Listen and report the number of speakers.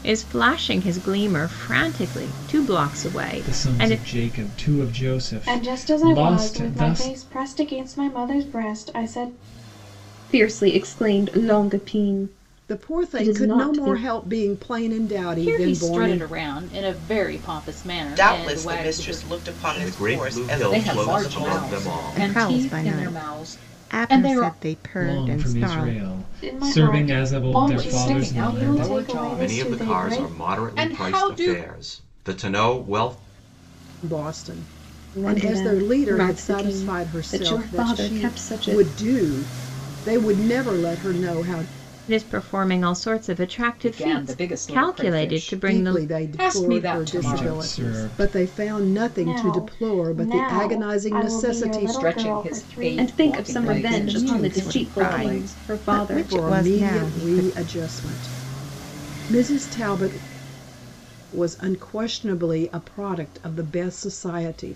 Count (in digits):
10